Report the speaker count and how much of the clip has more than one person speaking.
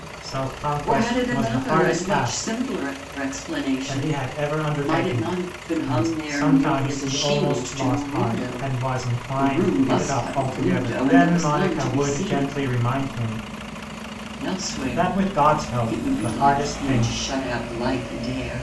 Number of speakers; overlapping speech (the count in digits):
2, about 67%